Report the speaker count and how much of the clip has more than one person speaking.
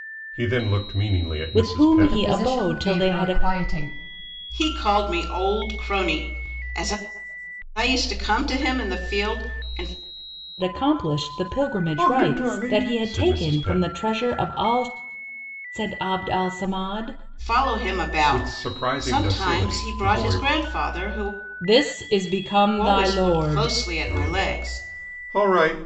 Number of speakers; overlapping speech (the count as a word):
four, about 28%